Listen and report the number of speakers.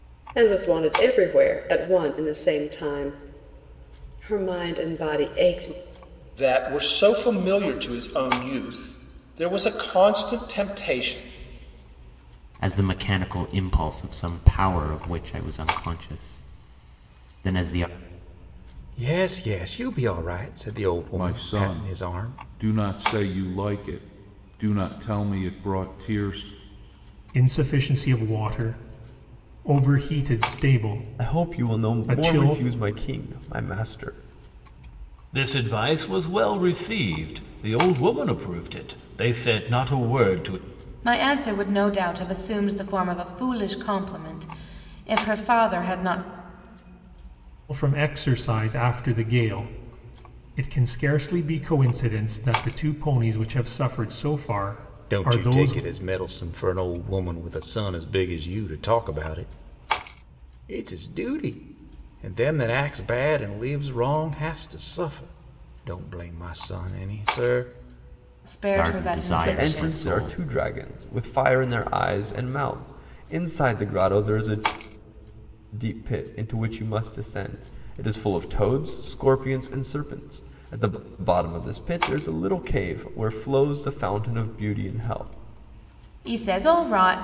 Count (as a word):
nine